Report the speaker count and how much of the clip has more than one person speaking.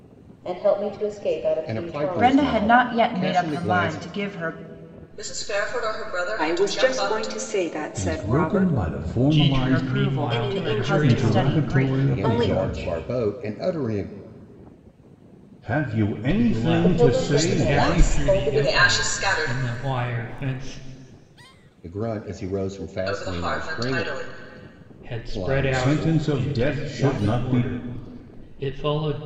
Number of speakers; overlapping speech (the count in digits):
7, about 50%